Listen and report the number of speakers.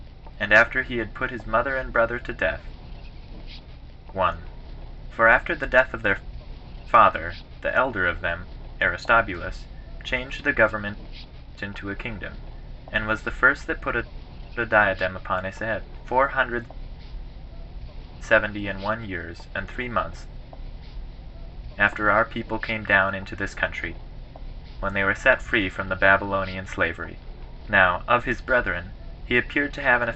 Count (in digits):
1